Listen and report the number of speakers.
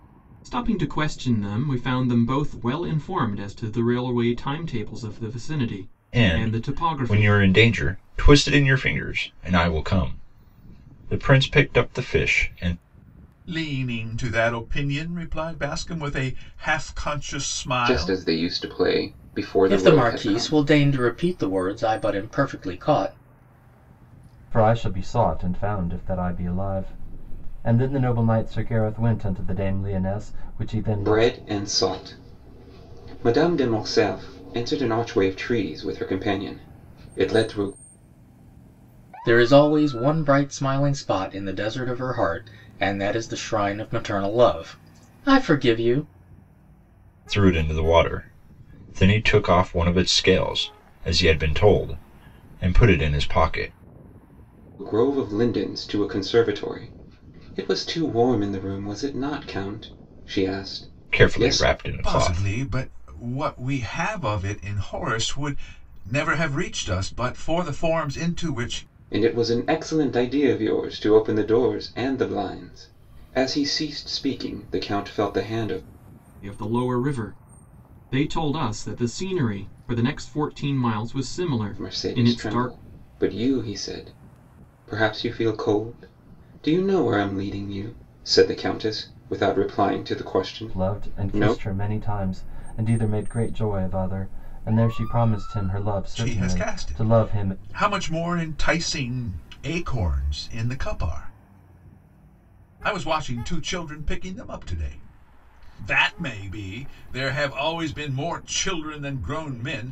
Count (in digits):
6